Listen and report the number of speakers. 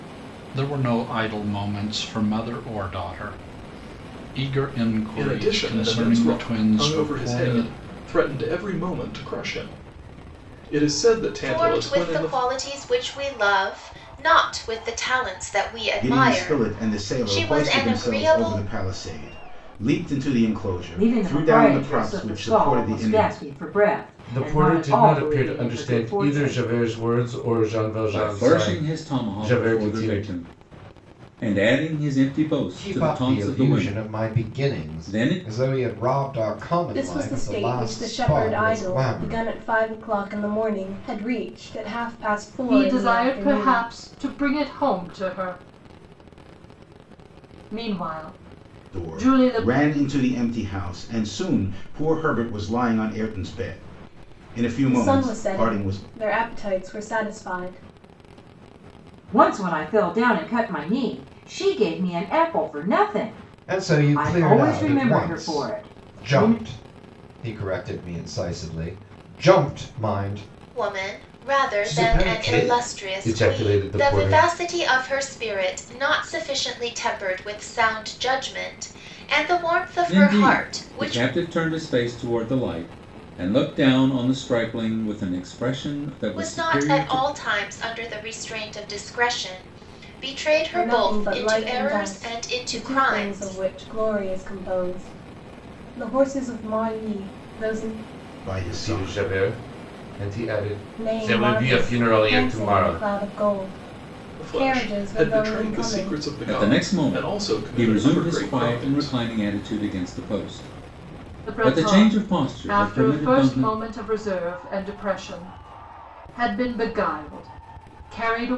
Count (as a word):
ten